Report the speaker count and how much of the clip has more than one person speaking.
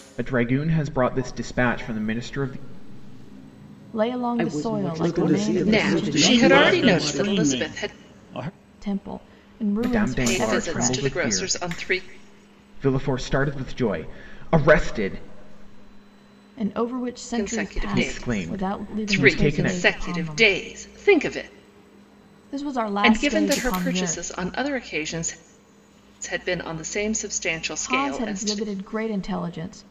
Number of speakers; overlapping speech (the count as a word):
six, about 36%